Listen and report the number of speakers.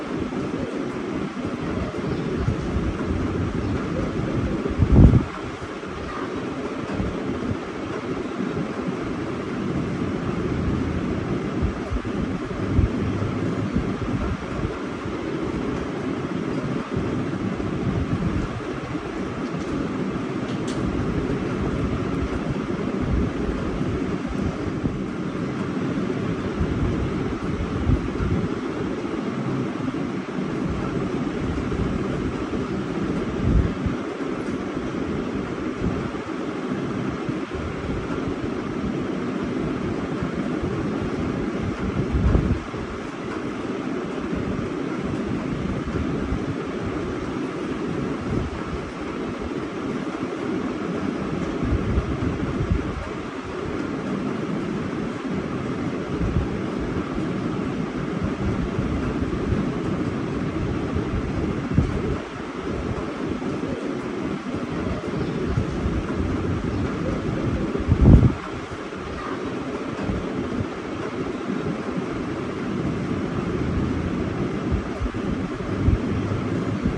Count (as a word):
zero